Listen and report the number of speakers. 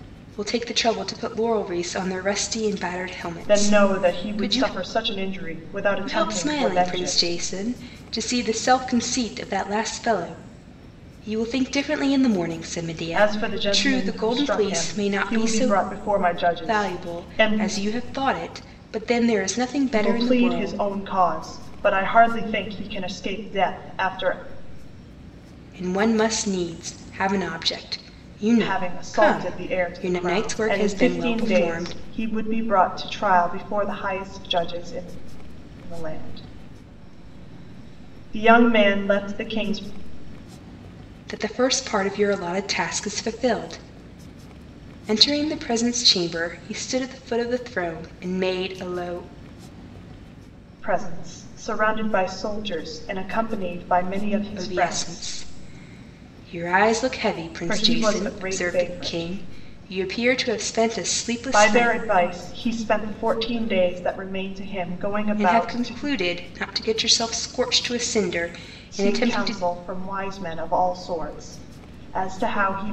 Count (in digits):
2